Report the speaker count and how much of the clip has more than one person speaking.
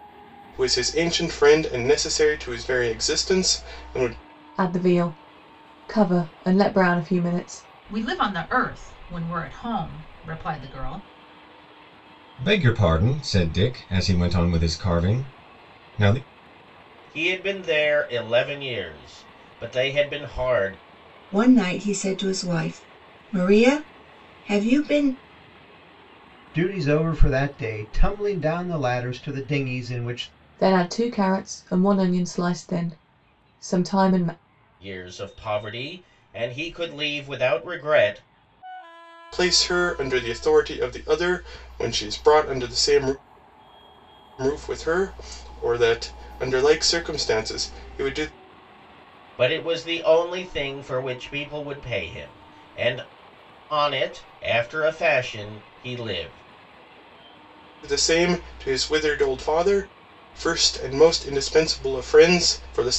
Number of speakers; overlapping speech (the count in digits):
7, no overlap